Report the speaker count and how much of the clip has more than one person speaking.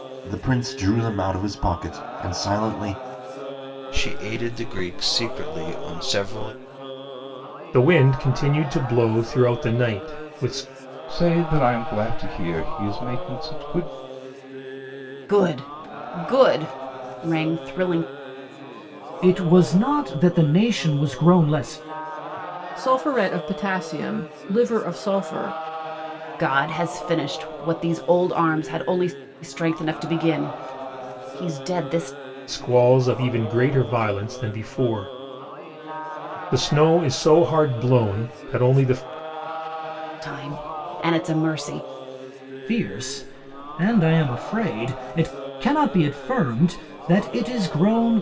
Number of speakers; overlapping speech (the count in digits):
7, no overlap